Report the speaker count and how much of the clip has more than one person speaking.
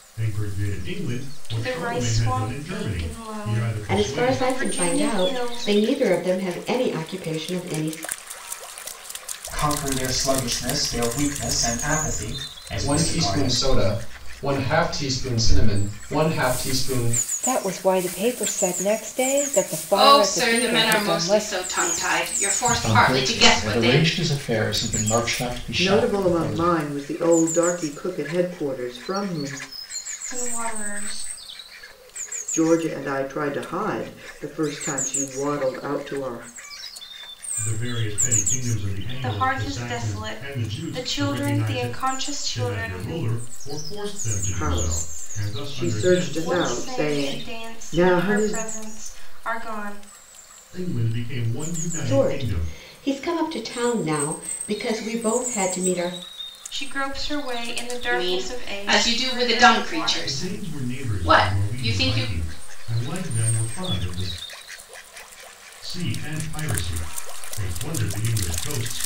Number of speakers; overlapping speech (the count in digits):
9, about 31%